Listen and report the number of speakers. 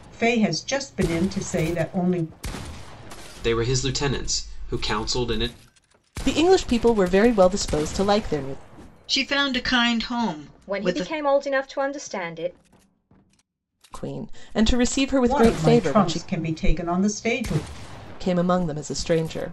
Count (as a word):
five